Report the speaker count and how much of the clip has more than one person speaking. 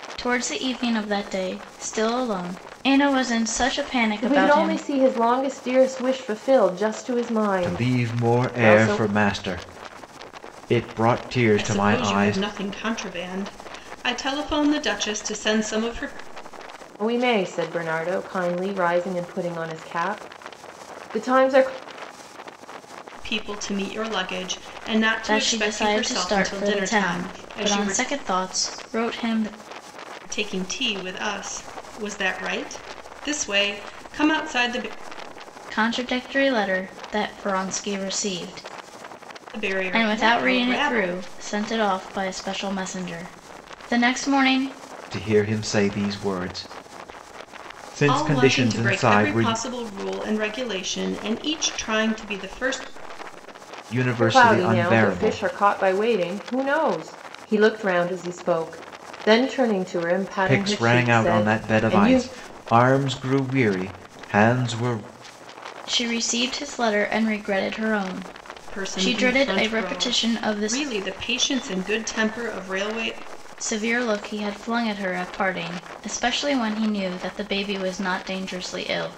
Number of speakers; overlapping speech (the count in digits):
4, about 18%